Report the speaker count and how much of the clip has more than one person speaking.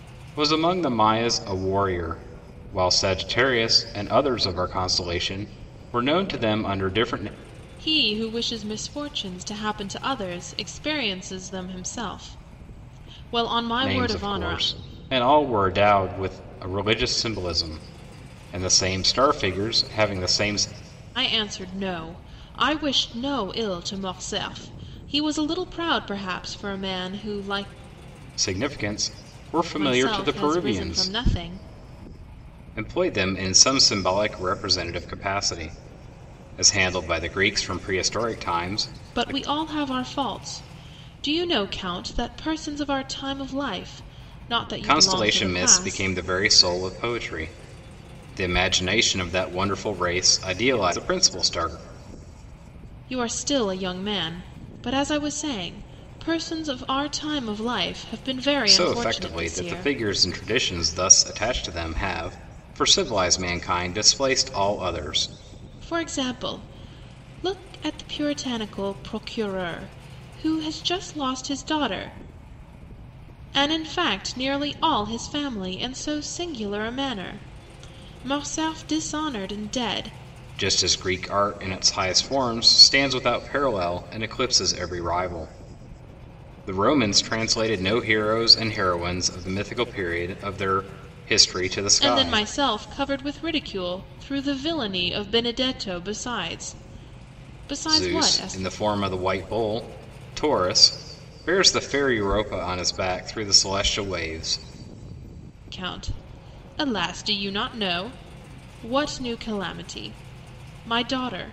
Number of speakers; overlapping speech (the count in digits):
2, about 6%